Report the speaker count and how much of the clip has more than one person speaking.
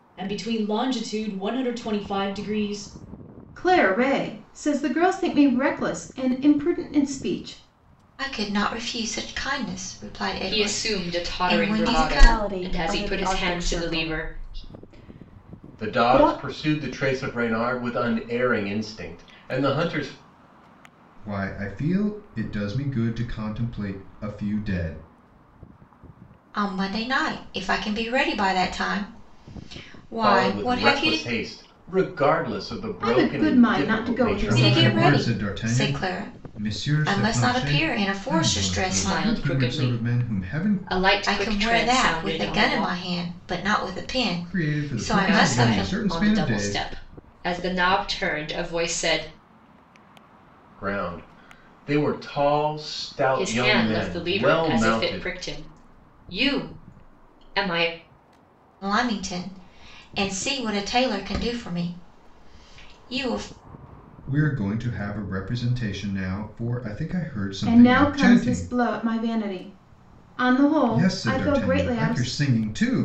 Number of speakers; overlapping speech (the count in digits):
7, about 30%